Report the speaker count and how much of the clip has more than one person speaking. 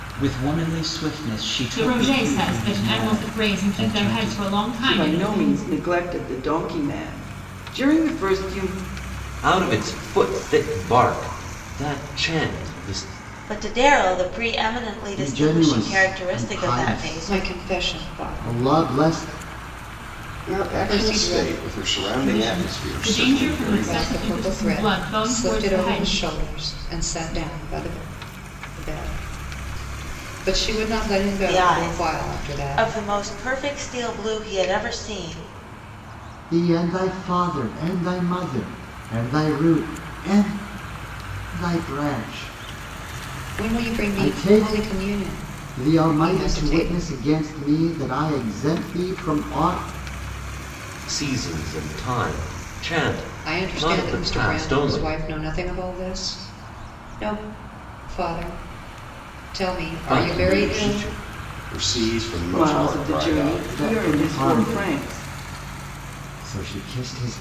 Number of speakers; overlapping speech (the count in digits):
8, about 34%